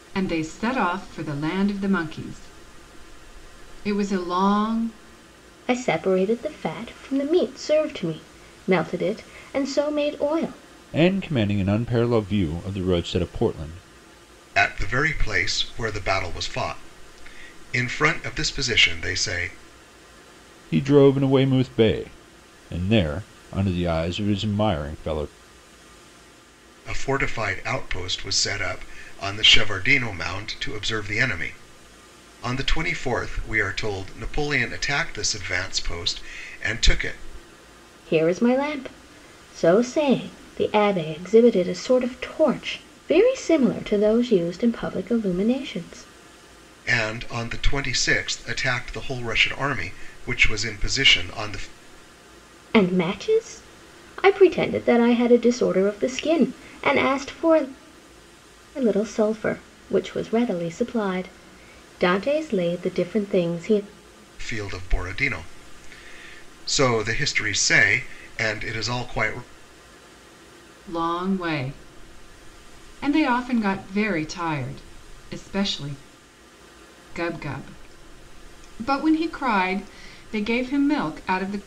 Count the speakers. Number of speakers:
four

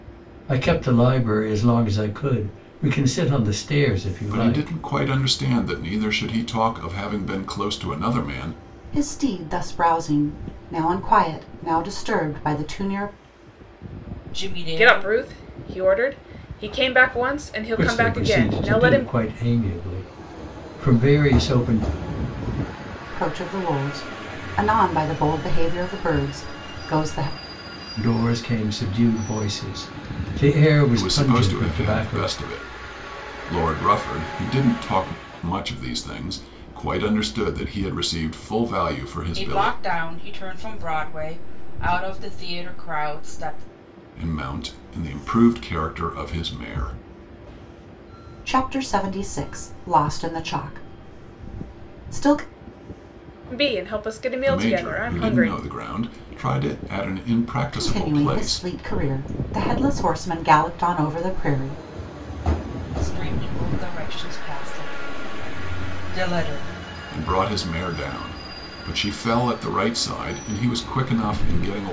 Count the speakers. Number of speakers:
five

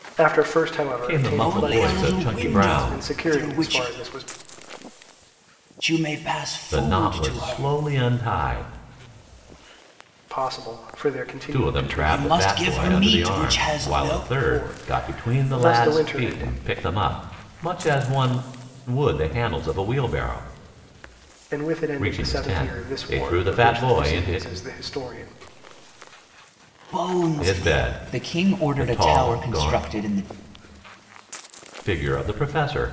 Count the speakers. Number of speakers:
three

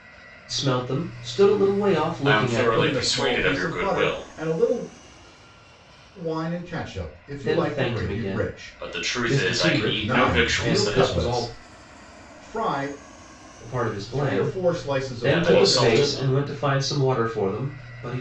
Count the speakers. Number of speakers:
three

